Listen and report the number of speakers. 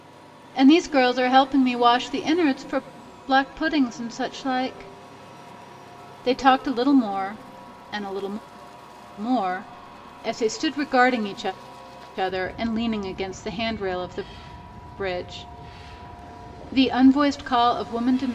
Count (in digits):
1